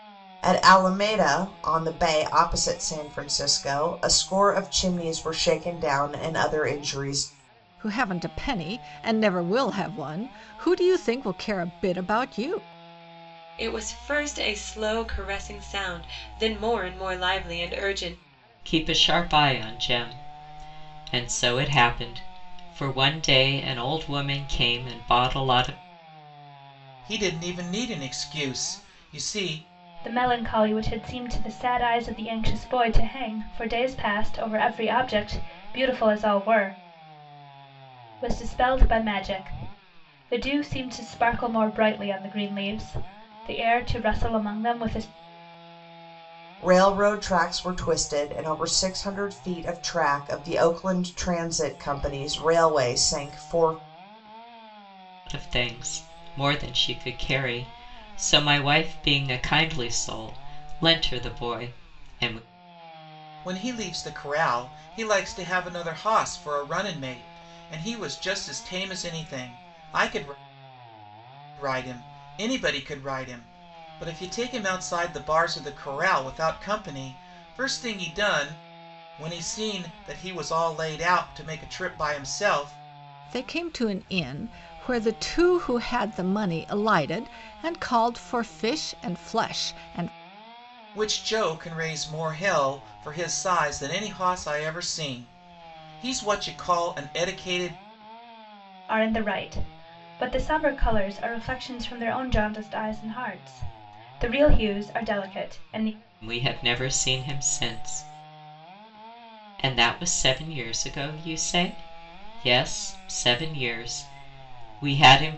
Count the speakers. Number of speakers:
six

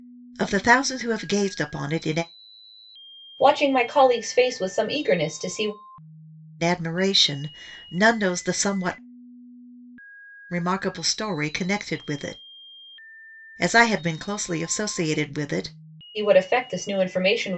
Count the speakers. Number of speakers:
two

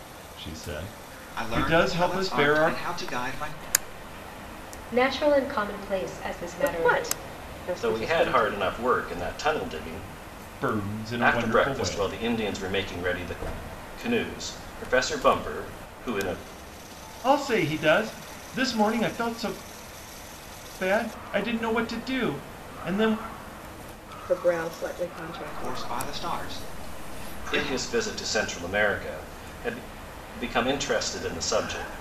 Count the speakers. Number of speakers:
five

